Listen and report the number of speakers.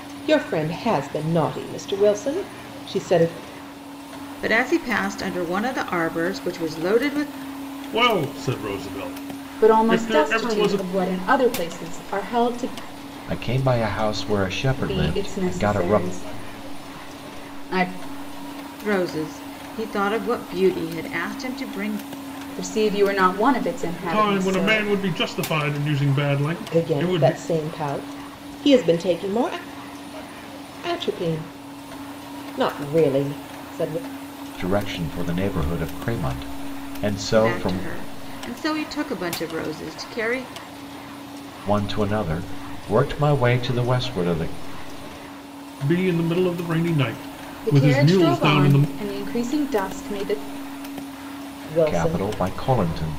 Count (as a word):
five